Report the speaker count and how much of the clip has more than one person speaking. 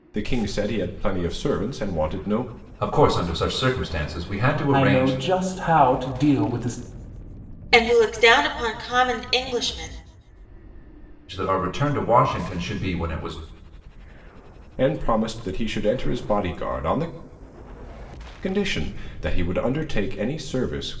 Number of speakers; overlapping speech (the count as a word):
four, about 2%